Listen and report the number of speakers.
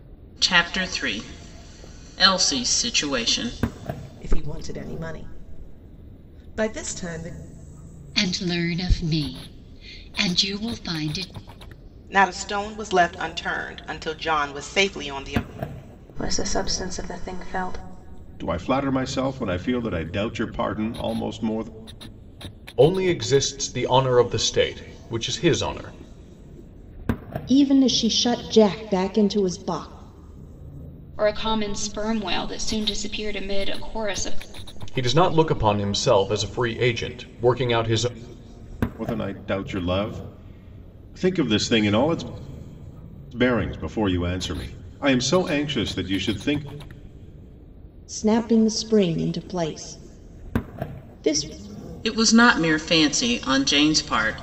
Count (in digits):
9